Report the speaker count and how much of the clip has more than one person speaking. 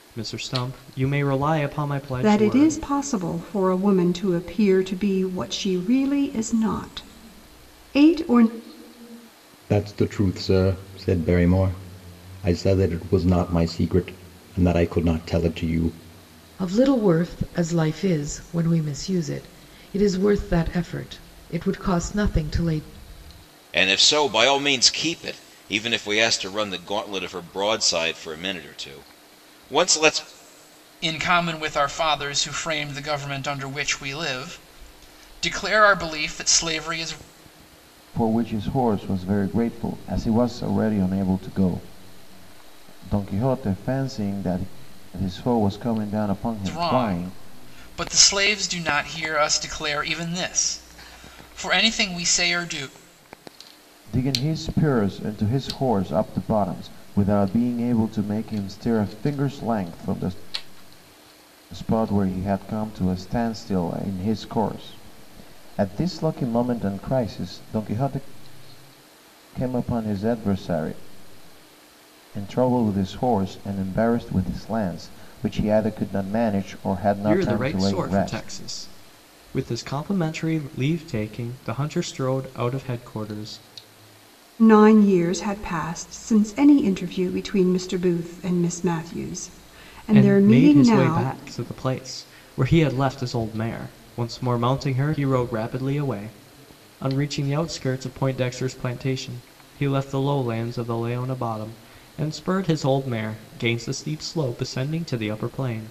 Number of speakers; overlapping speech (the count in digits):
7, about 4%